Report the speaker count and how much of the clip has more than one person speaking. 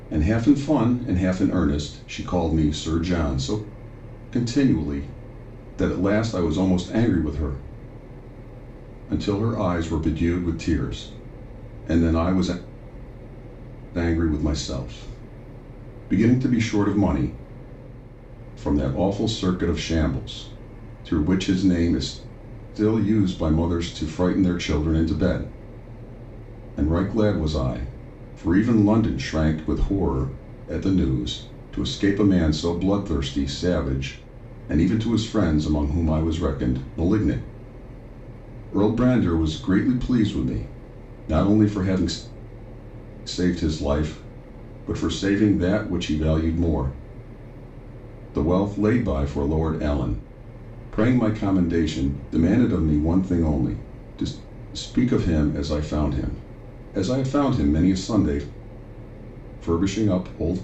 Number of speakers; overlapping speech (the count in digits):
1, no overlap